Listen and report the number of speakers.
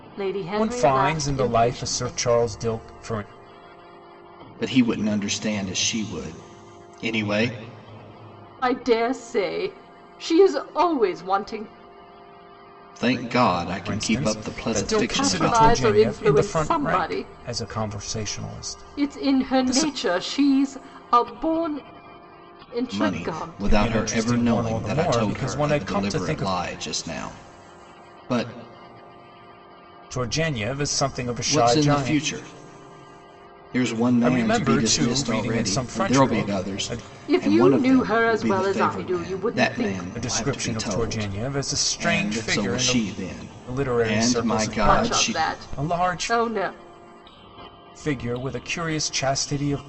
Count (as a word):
three